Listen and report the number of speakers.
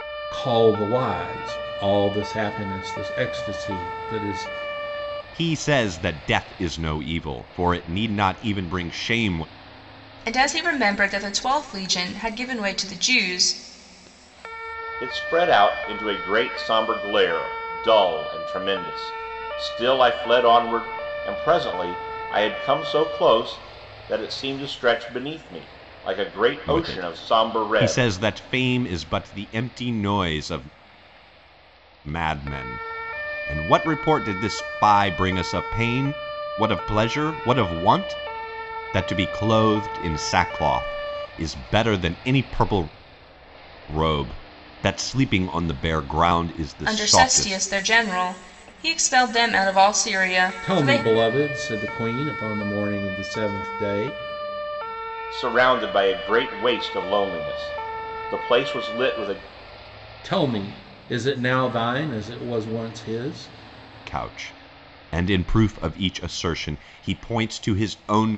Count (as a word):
four